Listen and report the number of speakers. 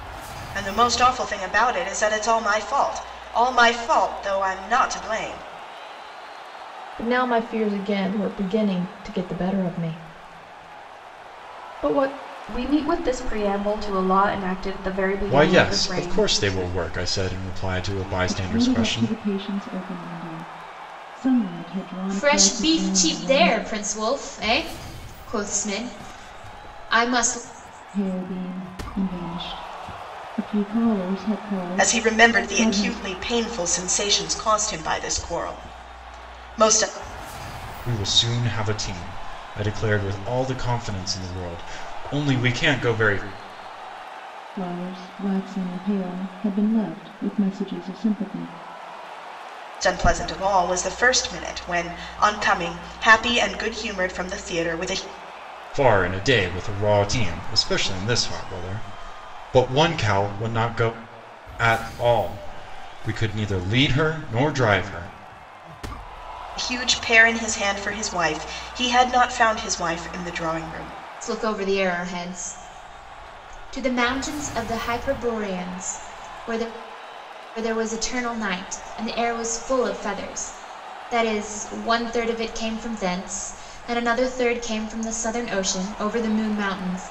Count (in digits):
6